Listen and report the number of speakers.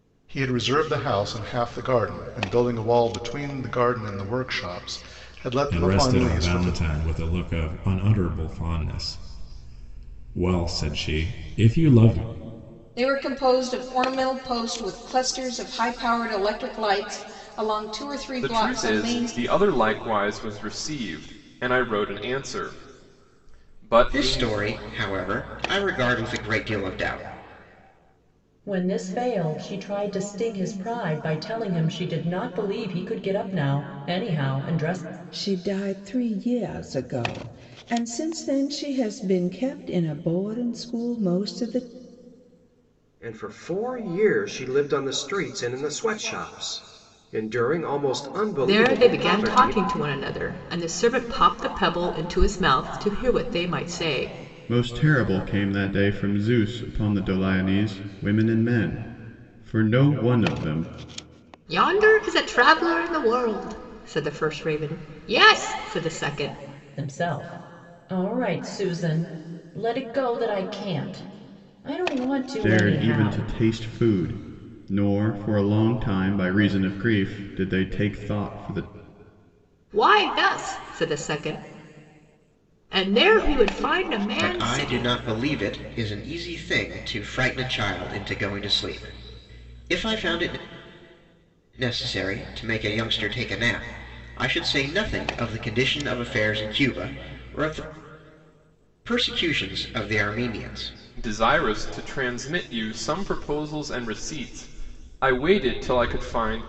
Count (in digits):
10